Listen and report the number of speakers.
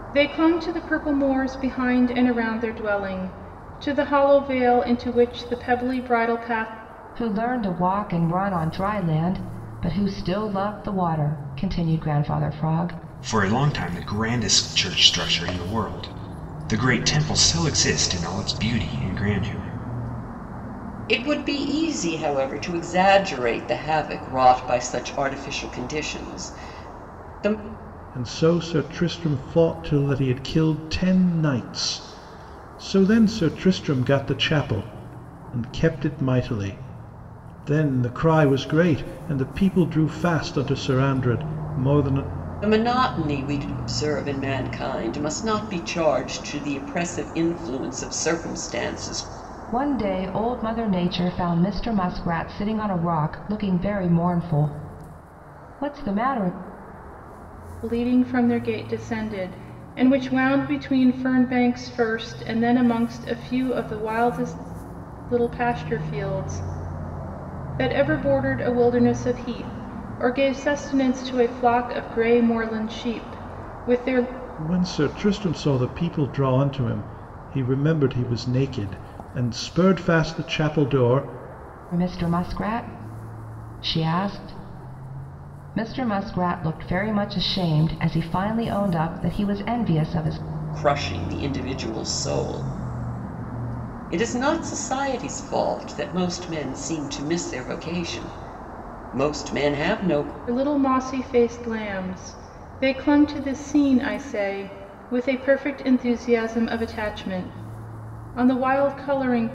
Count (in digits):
5